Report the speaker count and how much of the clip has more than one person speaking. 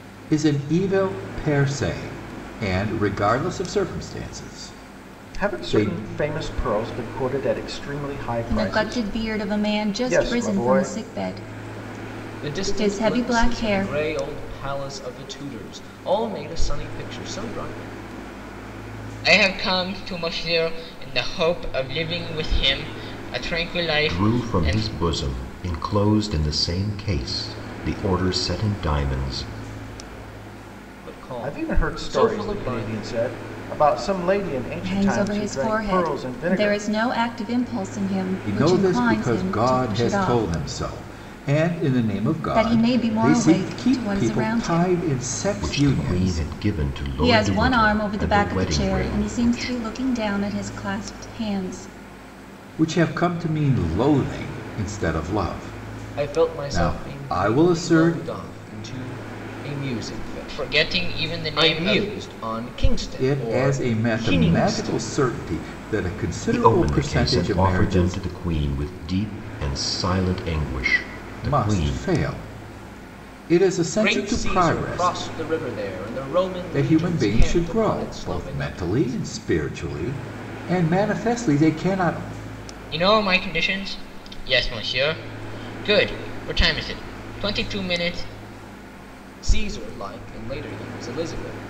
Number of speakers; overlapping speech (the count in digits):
6, about 32%